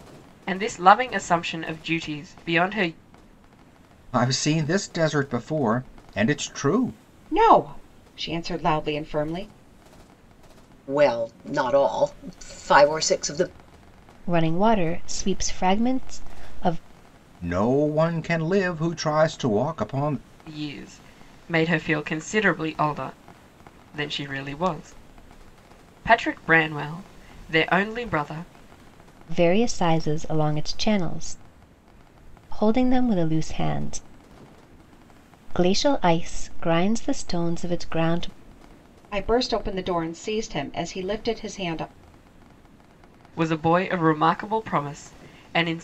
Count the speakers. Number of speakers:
five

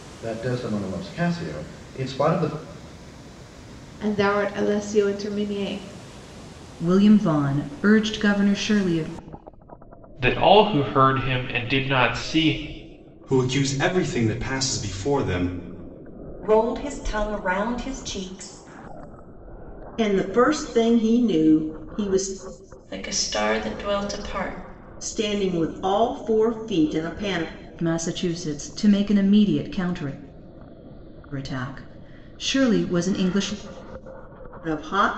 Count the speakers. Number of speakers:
eight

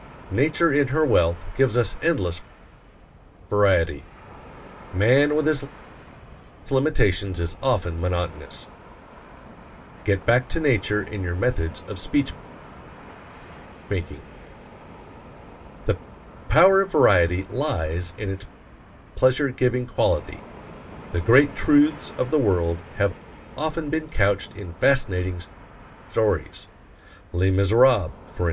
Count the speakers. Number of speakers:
one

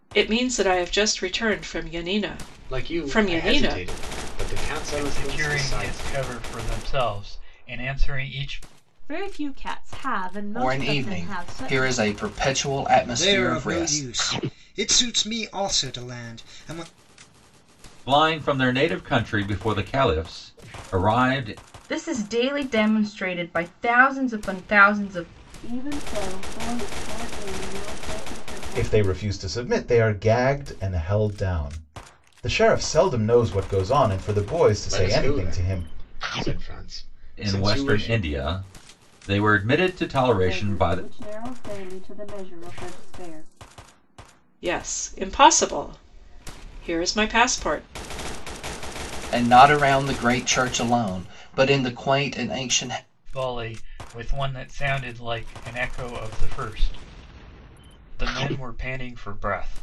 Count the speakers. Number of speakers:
ten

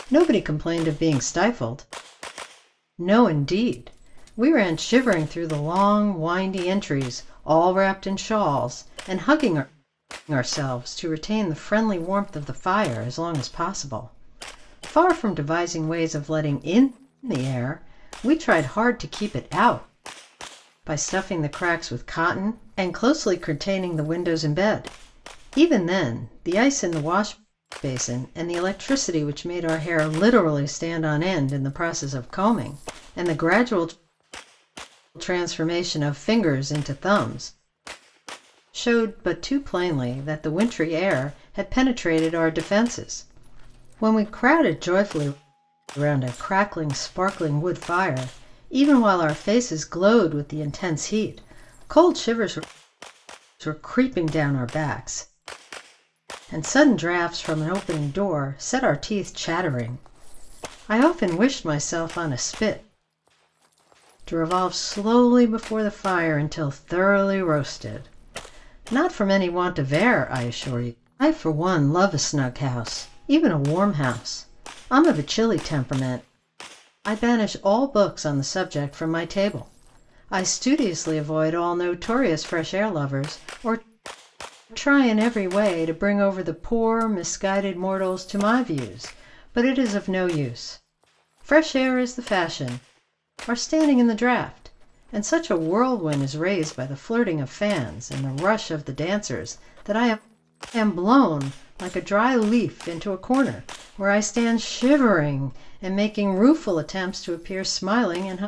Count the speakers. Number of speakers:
one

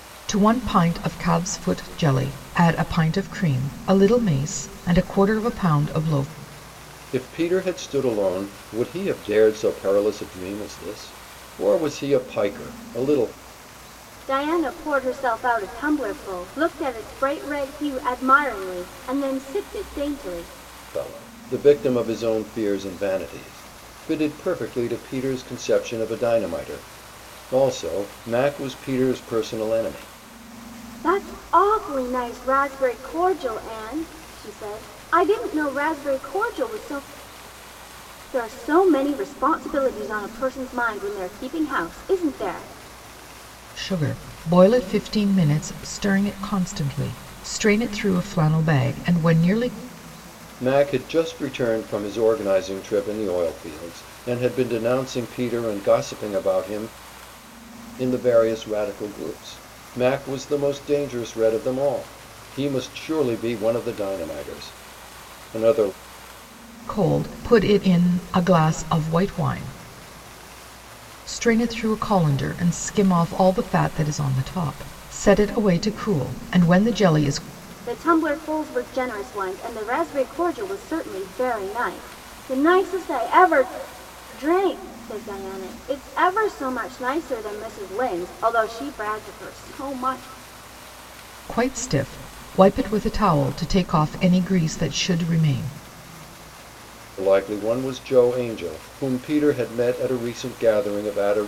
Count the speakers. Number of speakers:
three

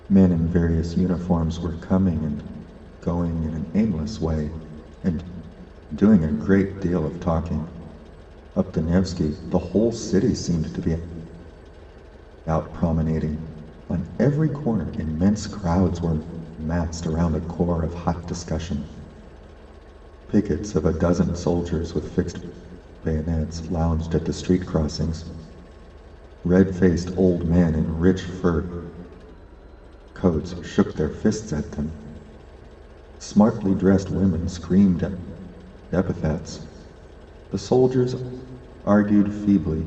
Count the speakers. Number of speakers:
one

